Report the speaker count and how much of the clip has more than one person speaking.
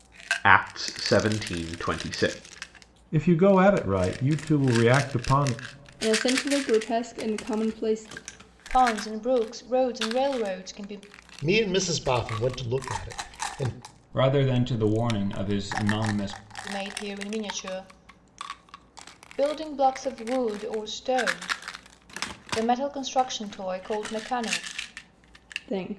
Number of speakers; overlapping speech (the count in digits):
6, no overlap